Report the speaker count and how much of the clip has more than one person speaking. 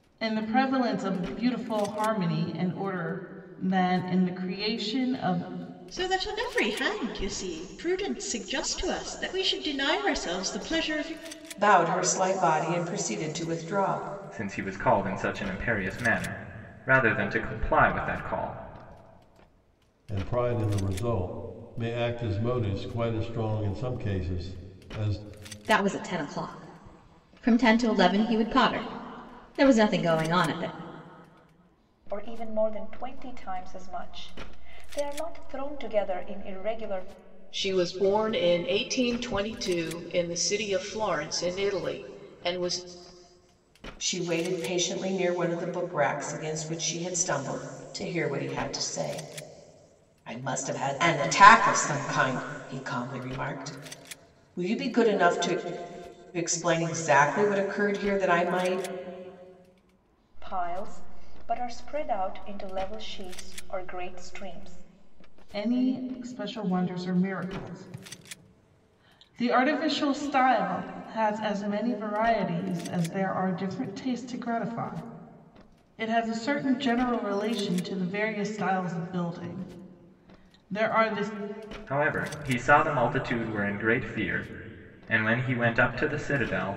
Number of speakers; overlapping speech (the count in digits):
8, no overlap